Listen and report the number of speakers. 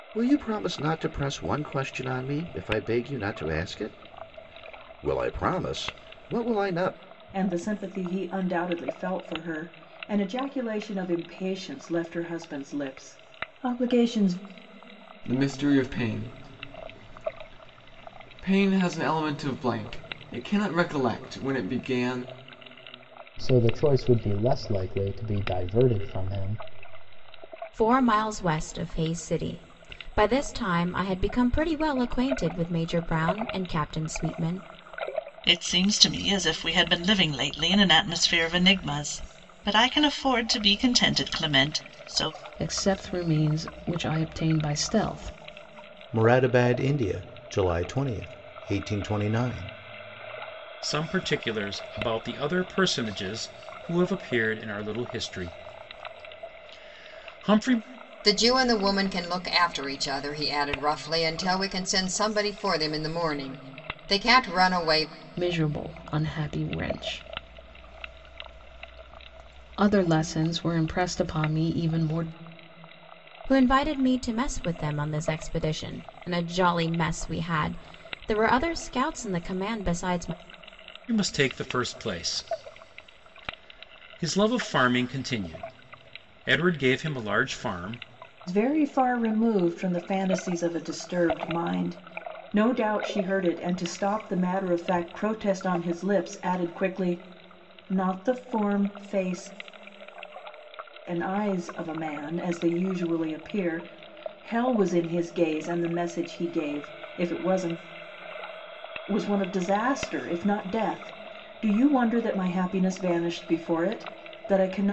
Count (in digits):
10